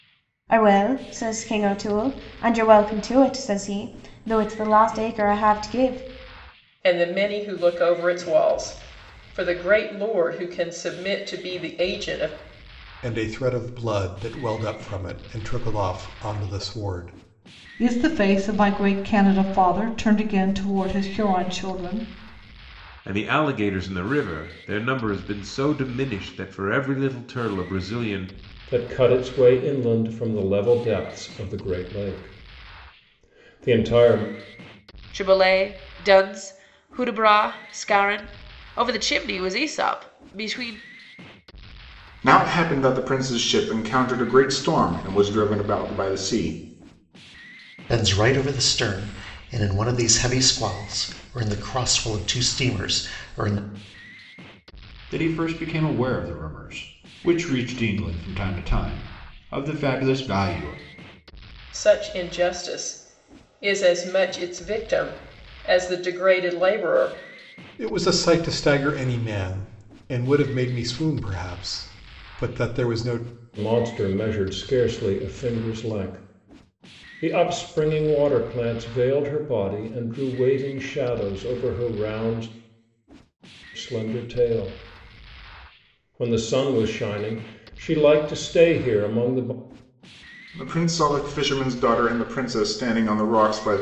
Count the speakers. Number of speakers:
ten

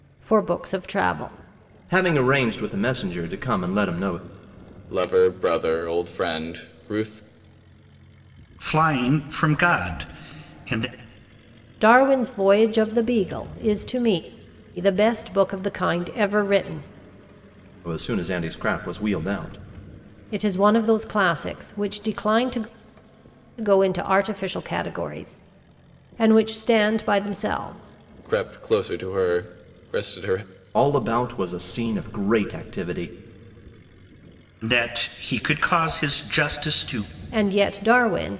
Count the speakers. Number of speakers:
four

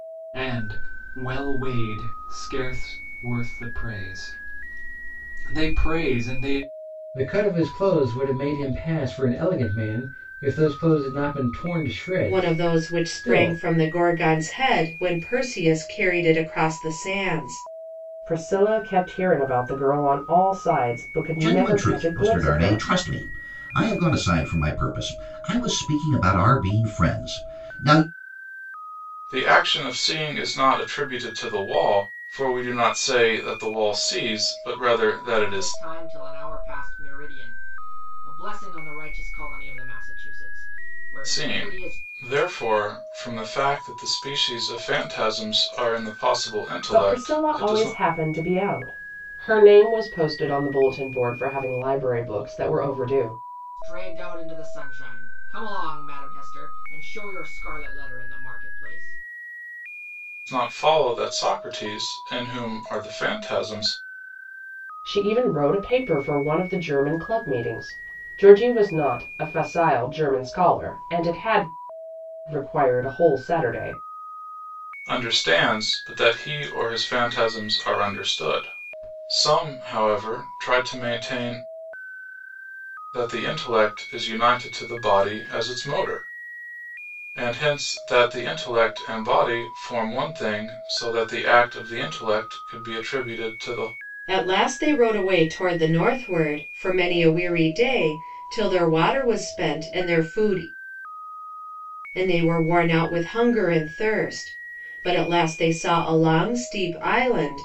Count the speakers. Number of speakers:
seven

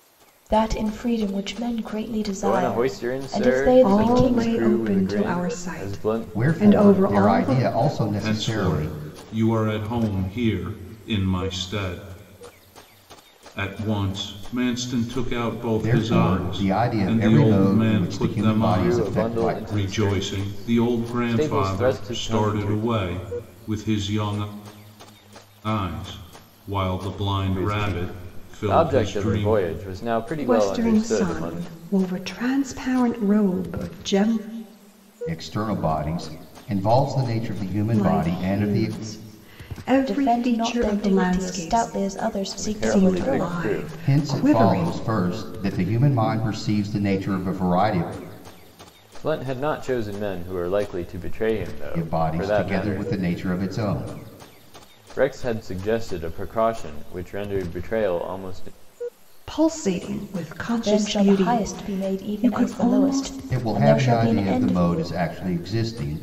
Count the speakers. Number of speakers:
five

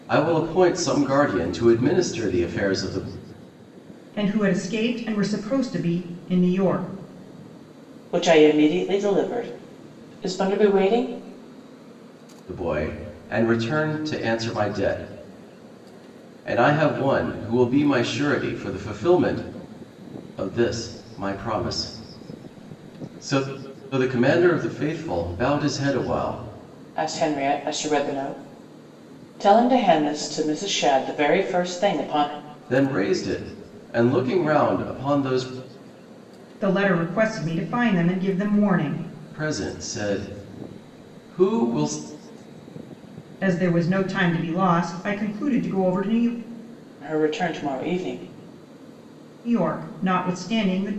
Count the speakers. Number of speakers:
three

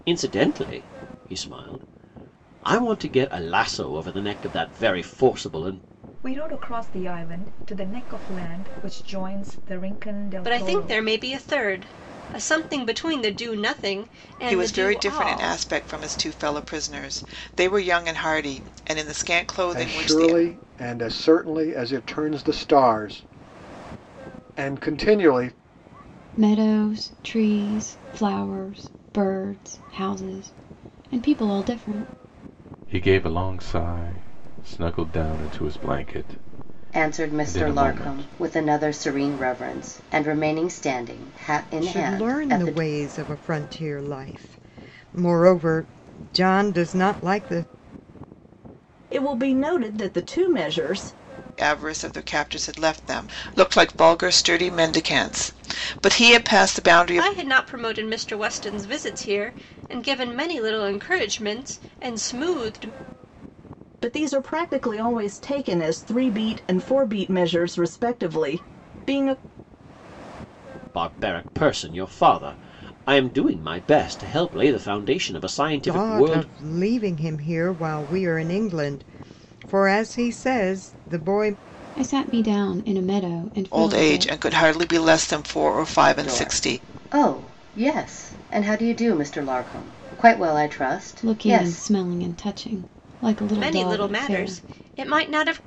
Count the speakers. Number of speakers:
ten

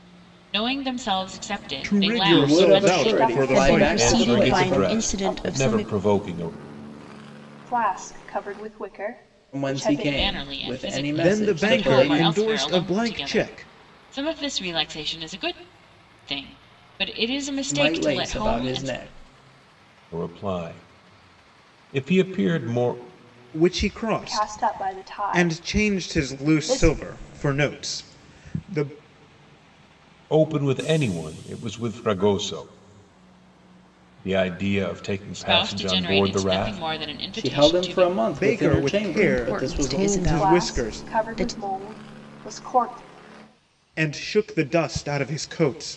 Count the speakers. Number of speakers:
six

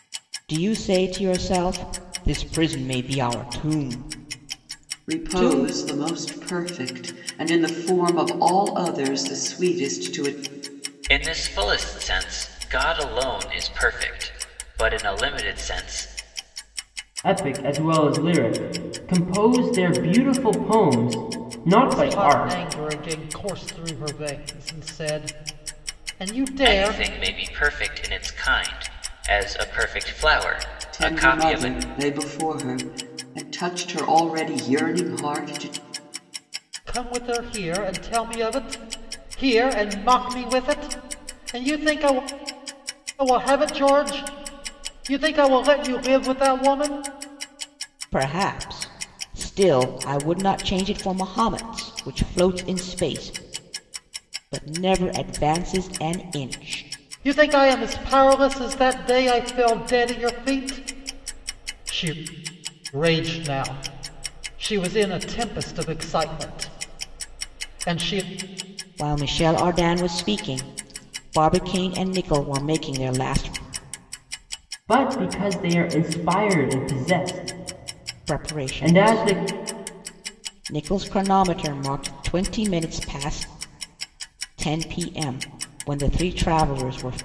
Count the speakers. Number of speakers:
five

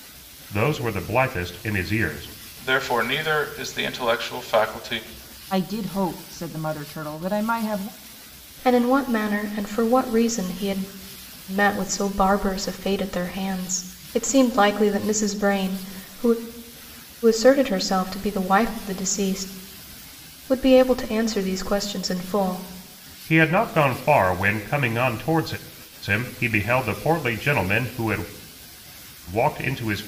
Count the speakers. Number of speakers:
four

